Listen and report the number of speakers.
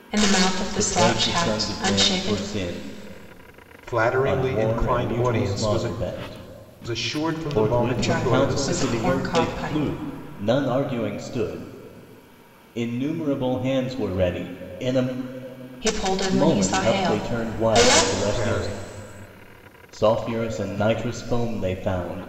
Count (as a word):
three